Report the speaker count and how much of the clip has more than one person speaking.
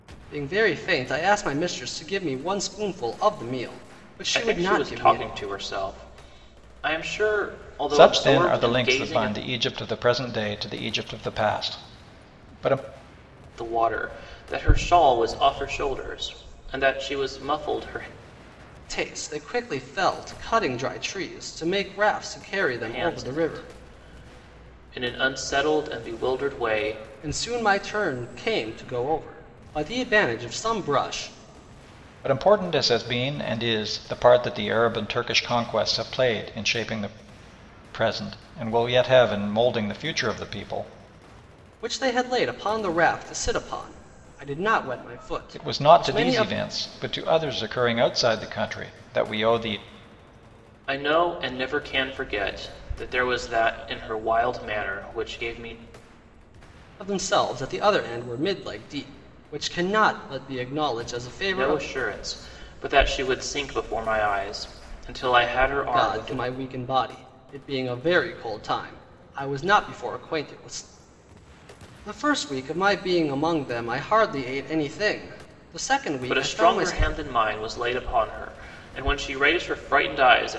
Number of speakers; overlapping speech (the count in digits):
3, about 8%